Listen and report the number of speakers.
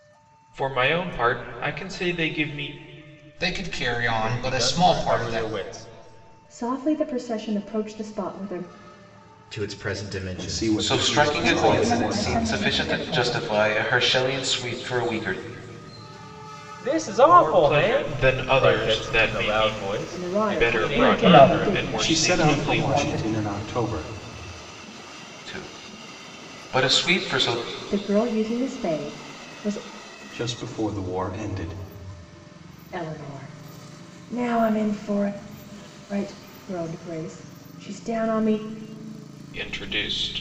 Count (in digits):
8